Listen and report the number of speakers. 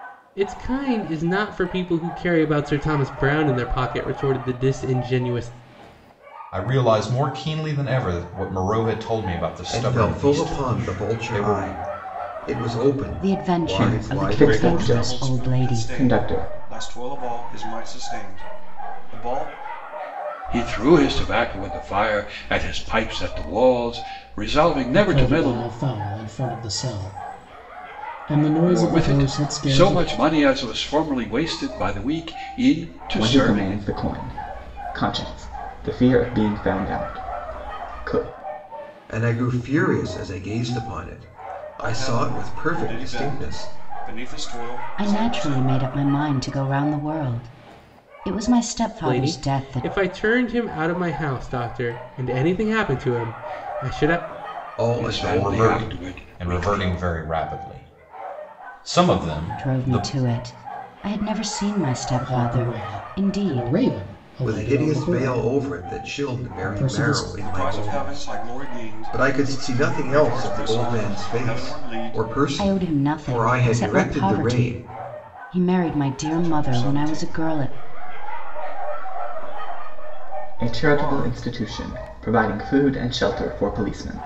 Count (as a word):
eight